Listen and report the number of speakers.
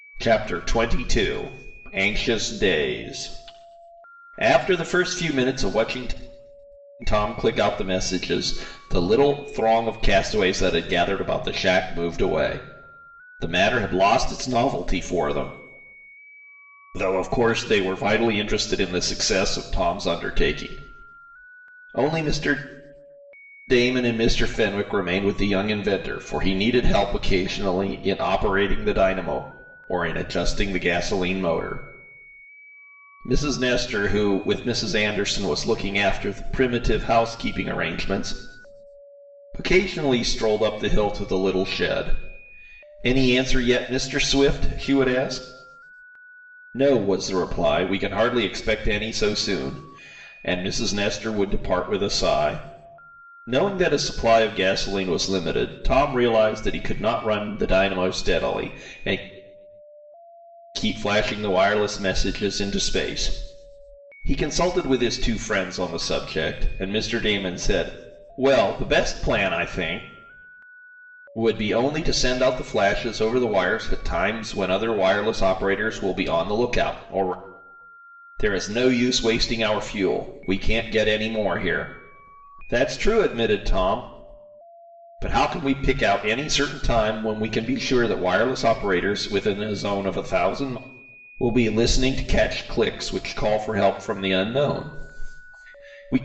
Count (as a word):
one